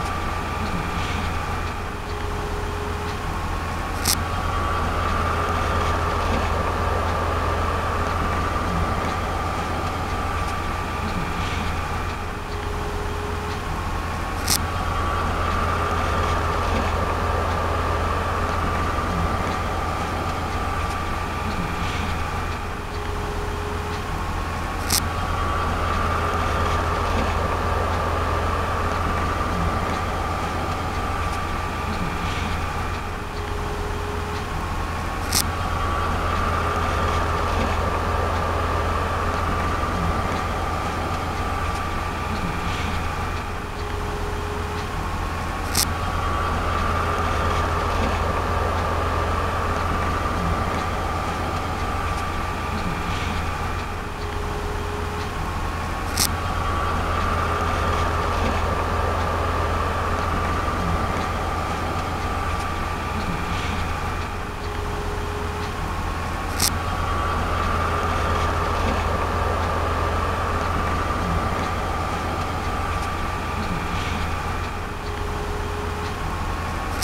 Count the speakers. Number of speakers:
0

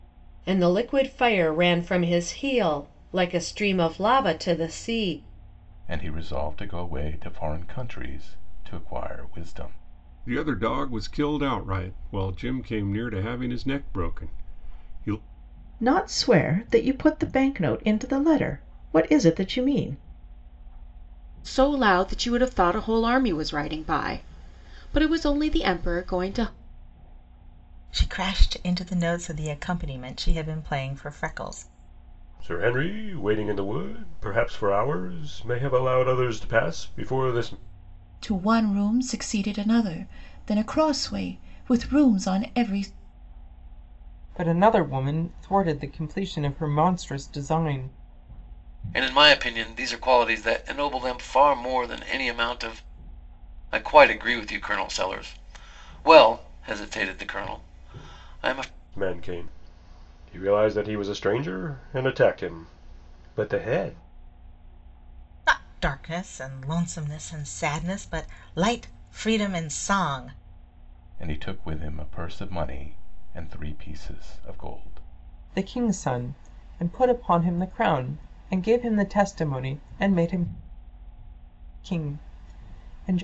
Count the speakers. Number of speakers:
10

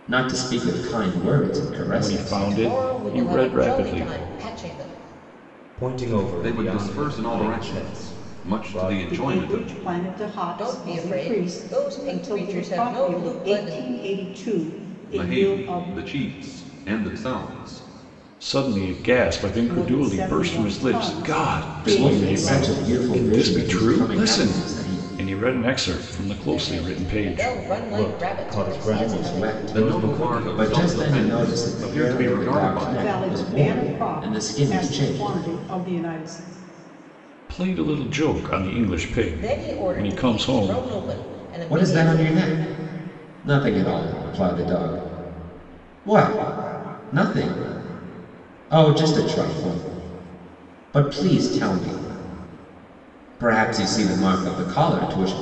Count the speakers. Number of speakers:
6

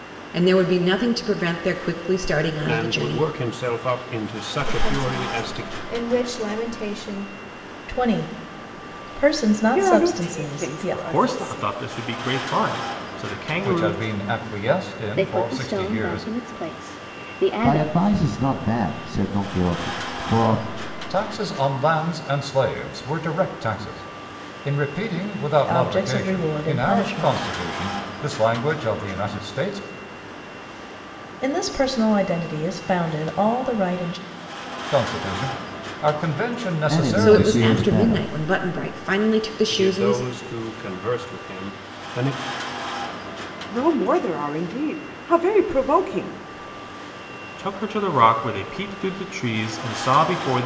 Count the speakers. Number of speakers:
9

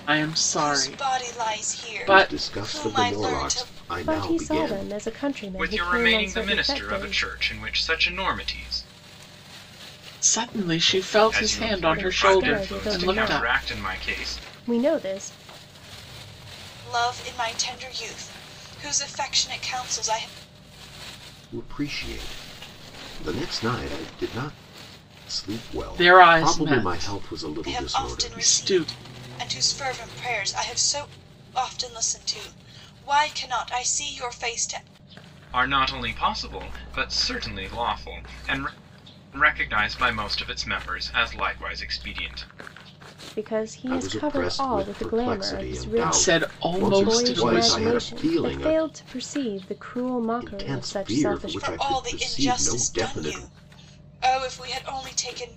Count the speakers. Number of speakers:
5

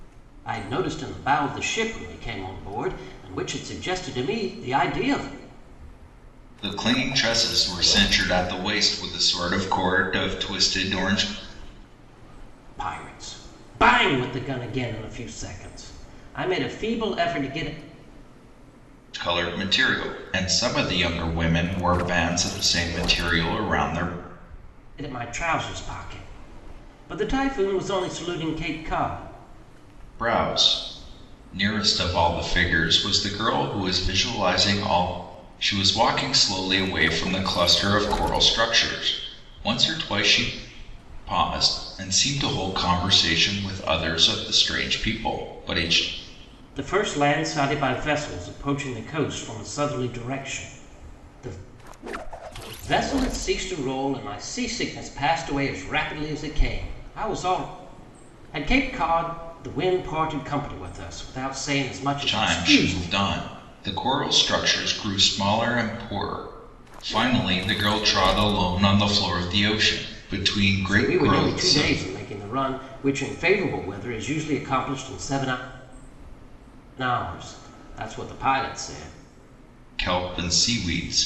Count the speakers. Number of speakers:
2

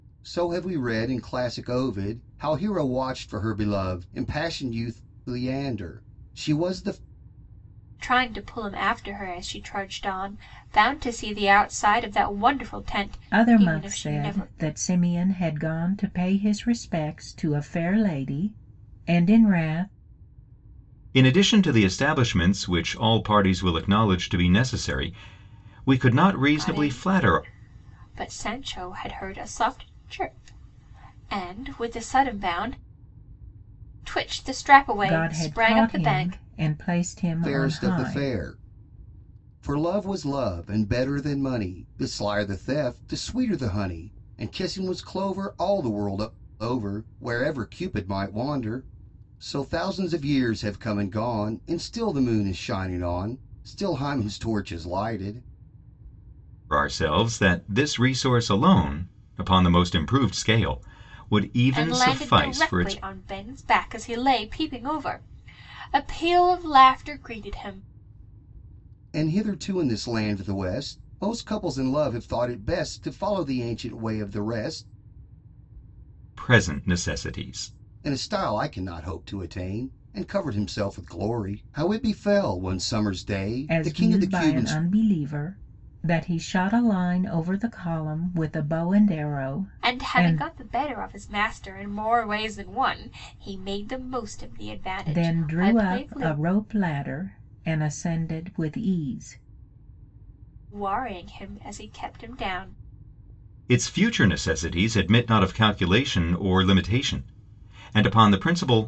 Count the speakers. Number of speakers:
4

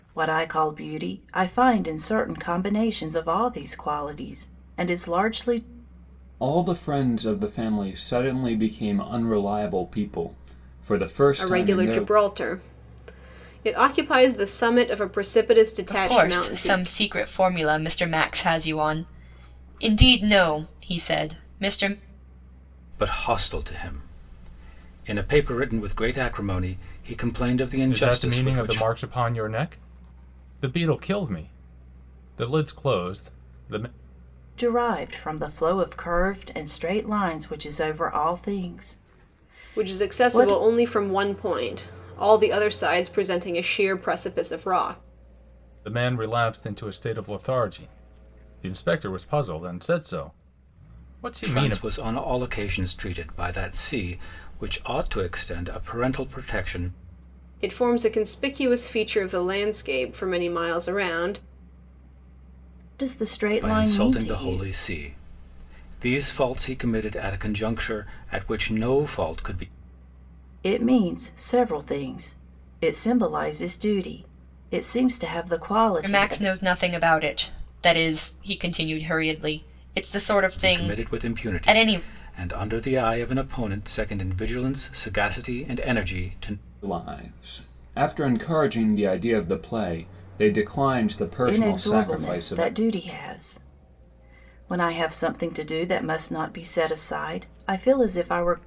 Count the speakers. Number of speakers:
6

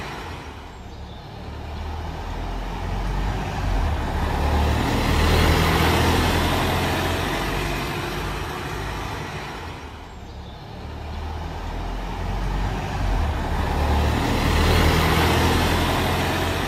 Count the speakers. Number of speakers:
0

